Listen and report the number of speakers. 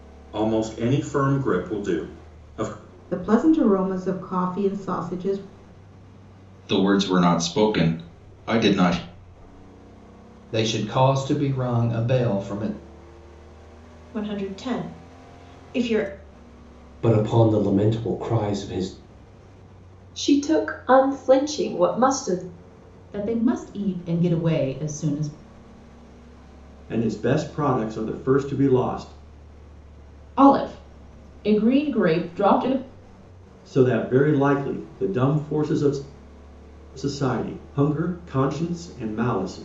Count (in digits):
10